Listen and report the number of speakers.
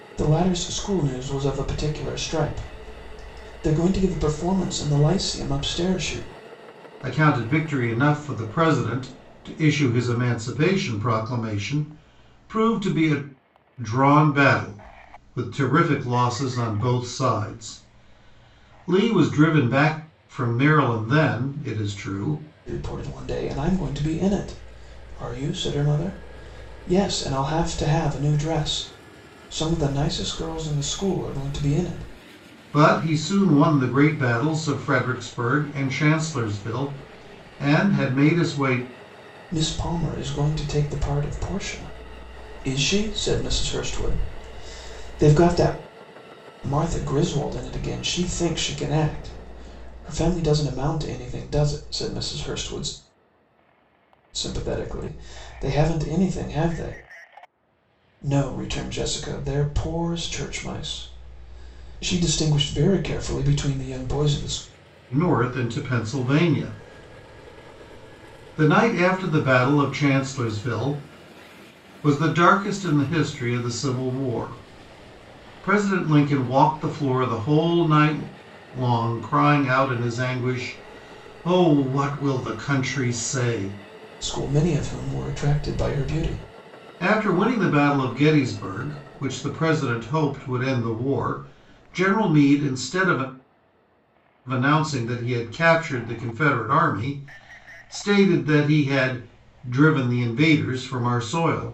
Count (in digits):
2